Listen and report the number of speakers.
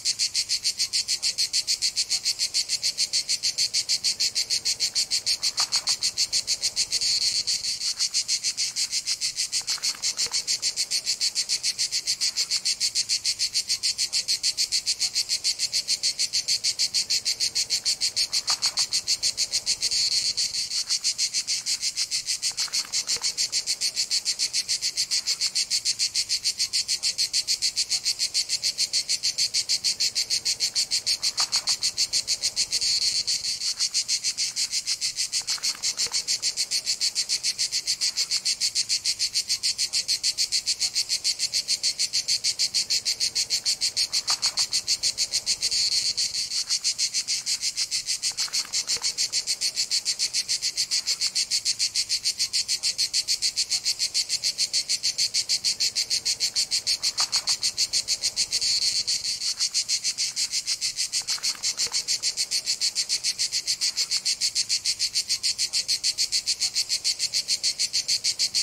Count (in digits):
0